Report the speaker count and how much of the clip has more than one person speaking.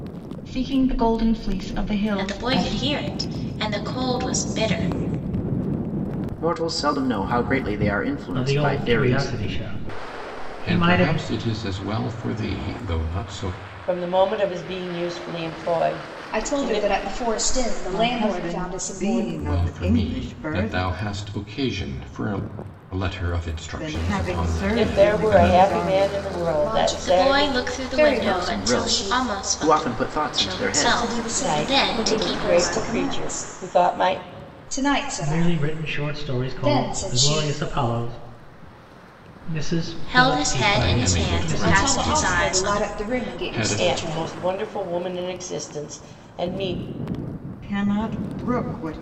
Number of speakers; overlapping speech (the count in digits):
8, about 44%